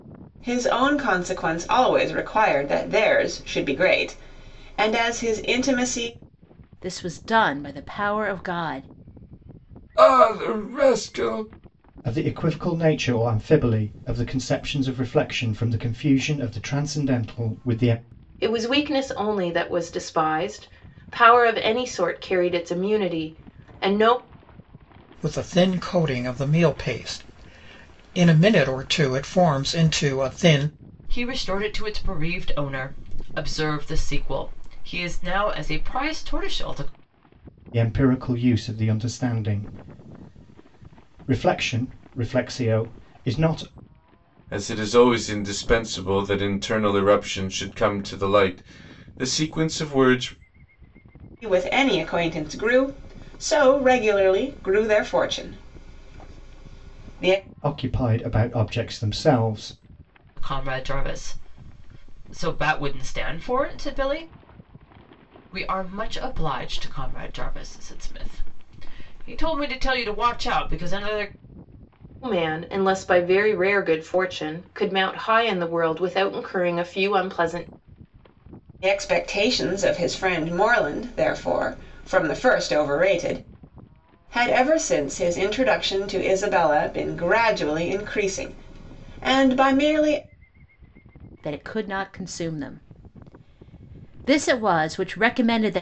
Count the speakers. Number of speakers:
7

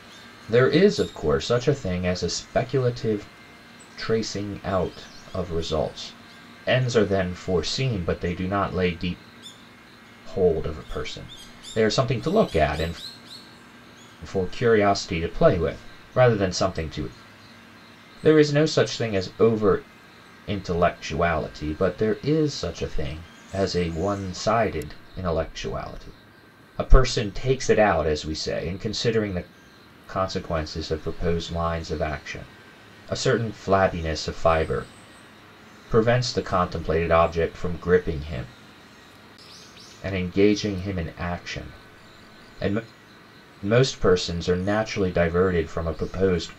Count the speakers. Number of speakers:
1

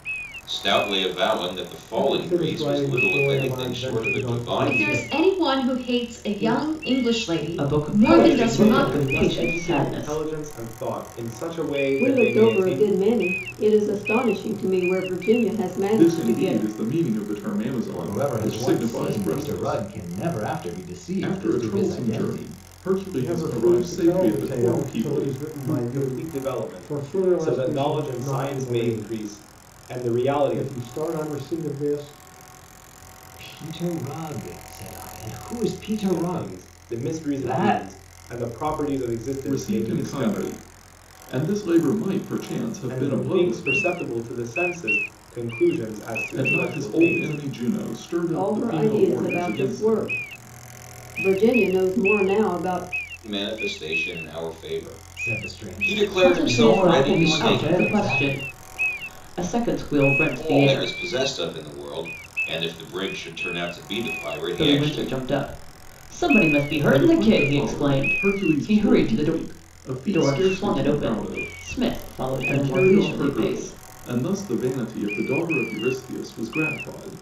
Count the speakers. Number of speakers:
8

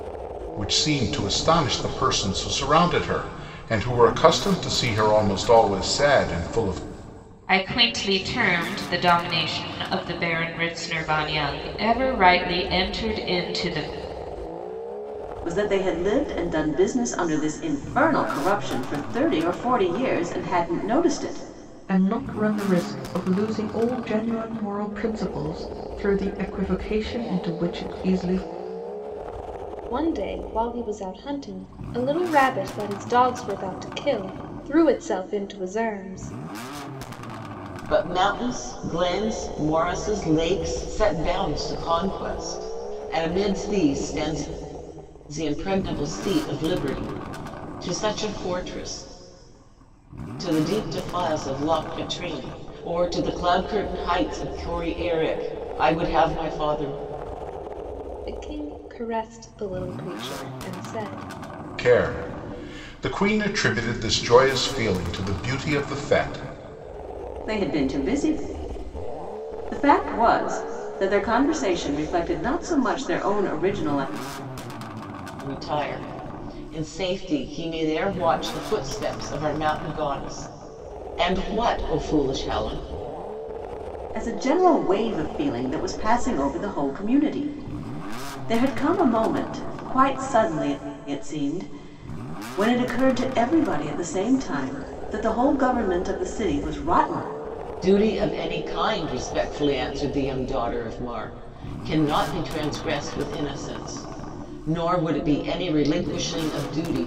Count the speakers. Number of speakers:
6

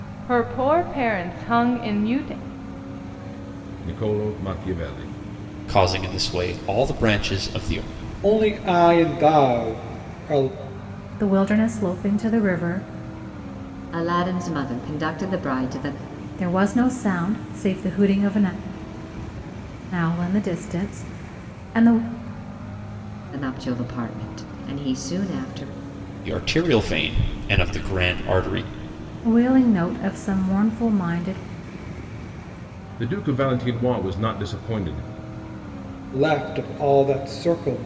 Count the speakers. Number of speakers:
6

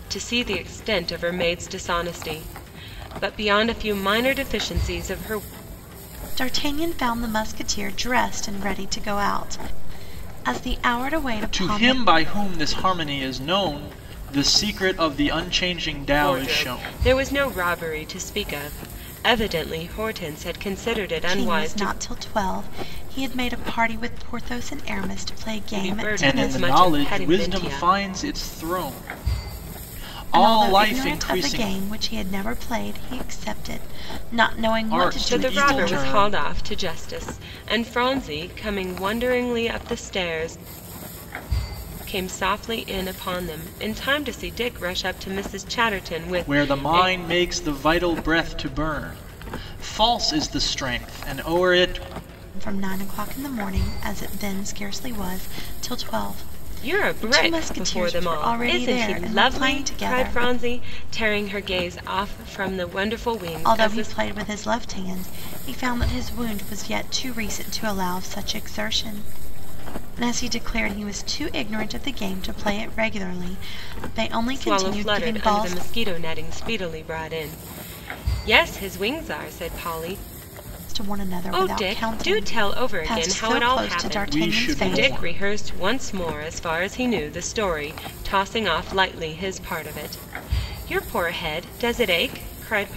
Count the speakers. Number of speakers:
3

